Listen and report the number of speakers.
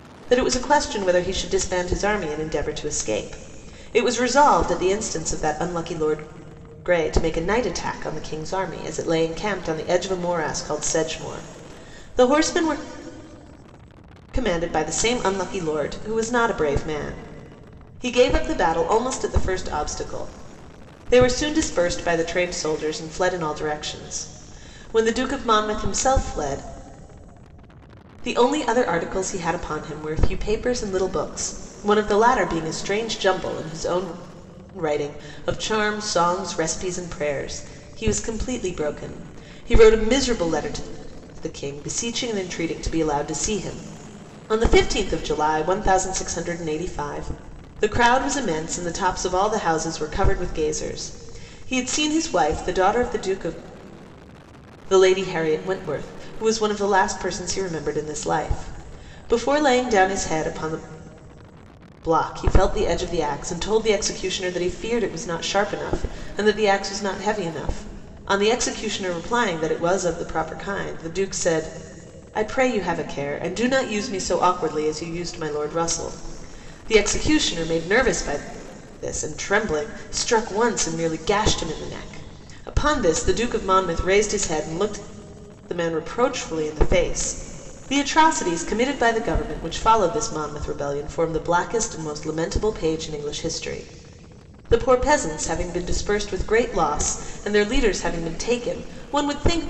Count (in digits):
1